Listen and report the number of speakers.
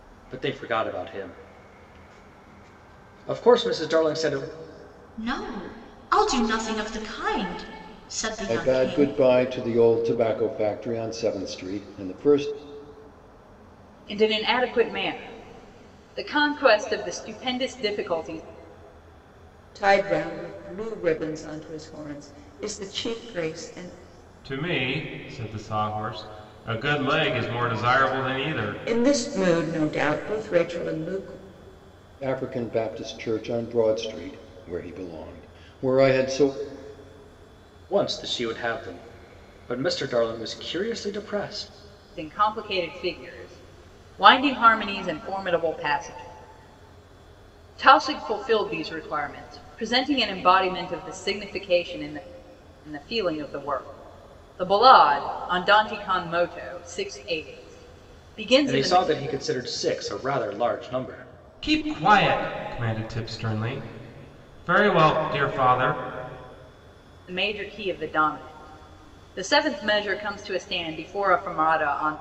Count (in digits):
6